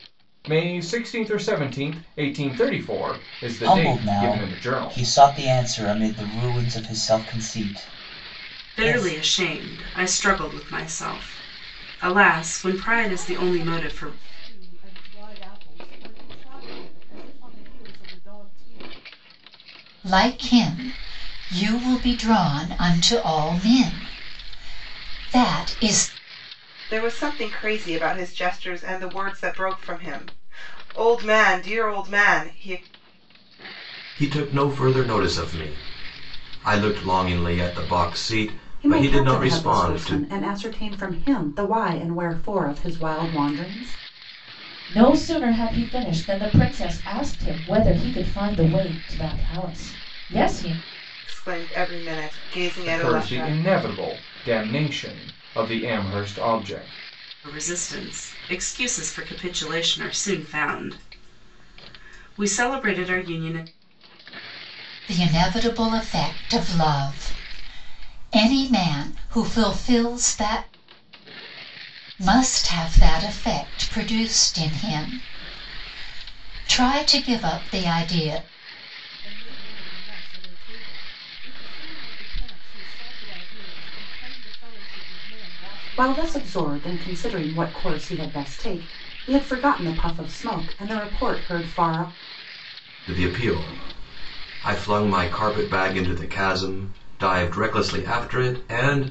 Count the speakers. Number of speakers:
nine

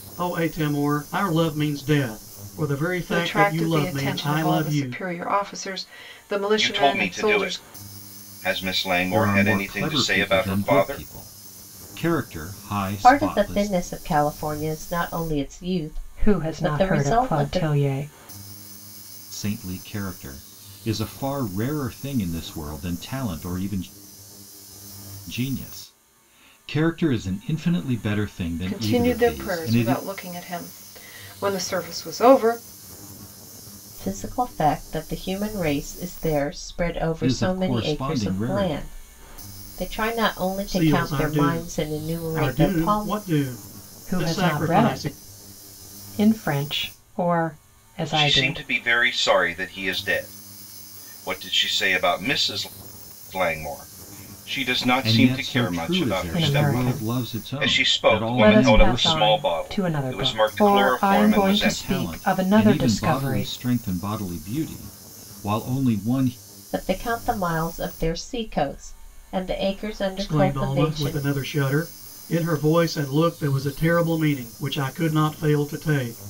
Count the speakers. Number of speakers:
six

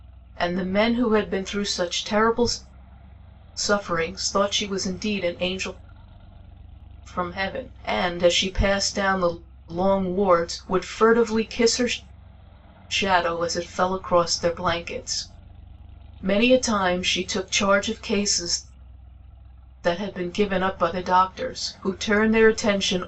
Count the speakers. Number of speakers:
one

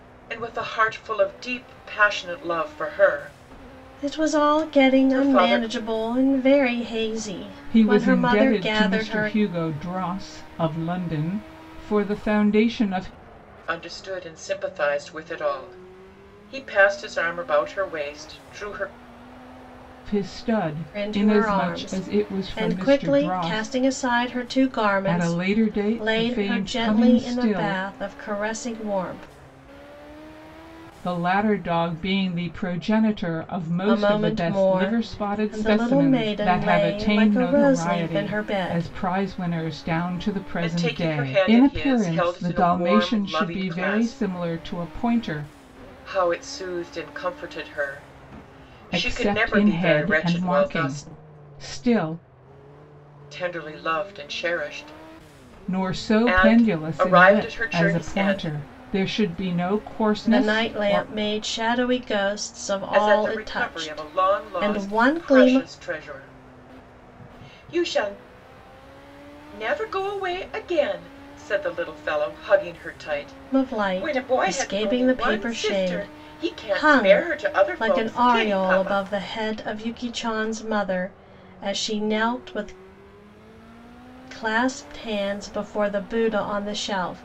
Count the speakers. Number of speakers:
three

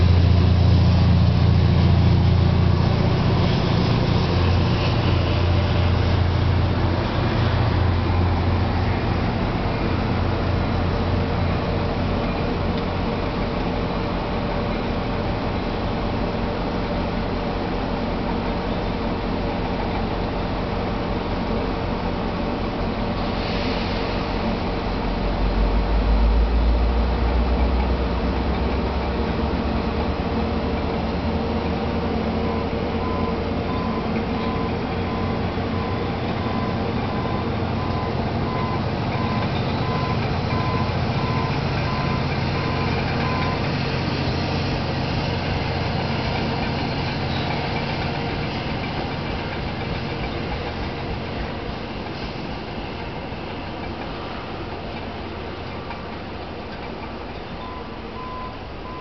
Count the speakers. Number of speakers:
zero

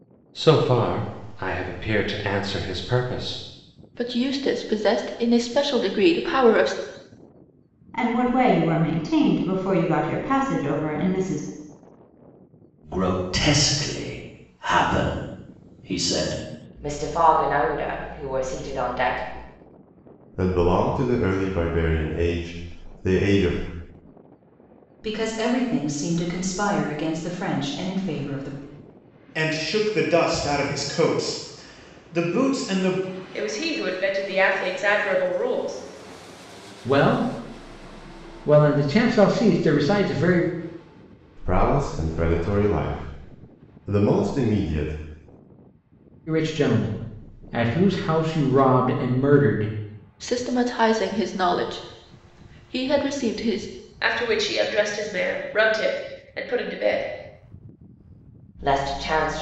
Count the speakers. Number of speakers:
ten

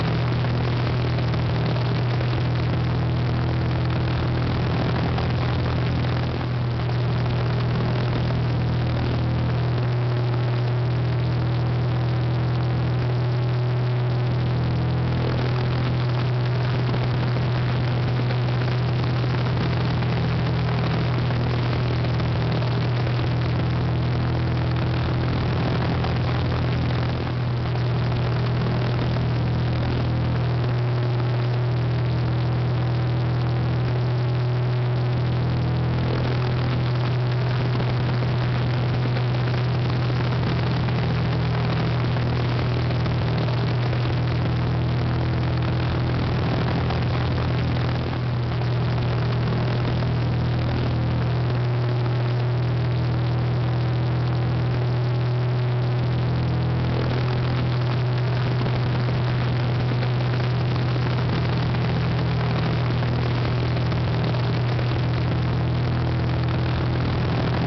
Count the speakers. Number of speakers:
zero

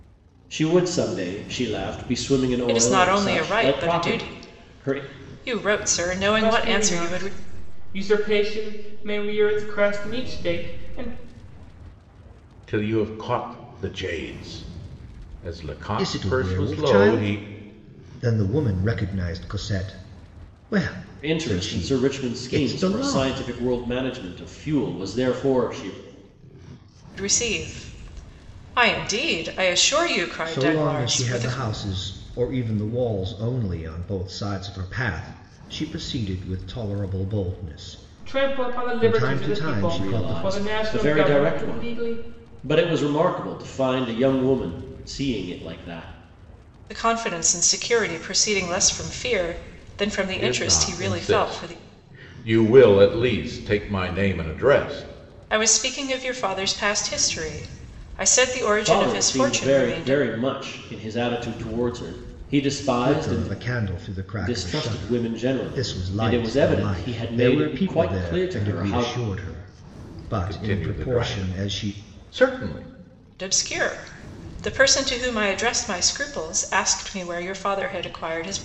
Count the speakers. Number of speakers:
five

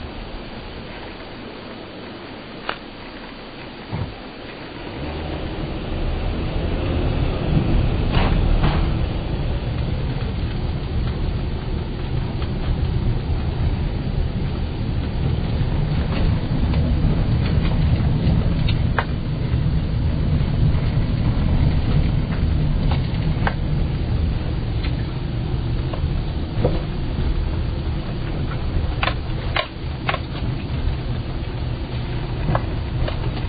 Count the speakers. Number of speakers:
zero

